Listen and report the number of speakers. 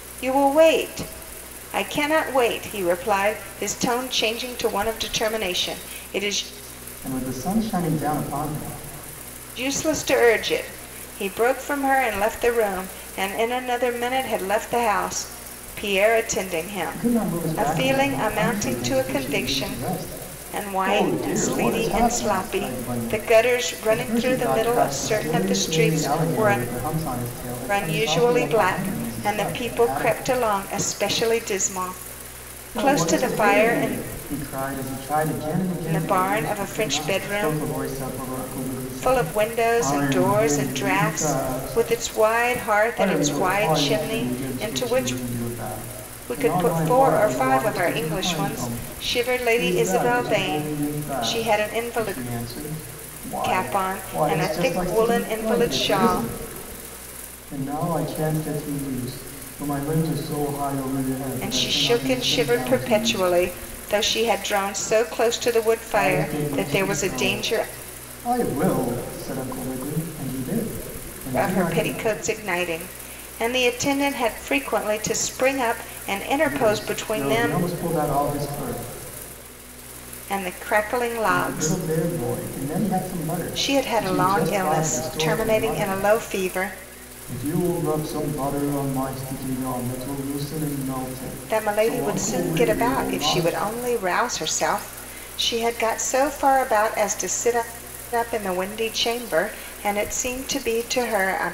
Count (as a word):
two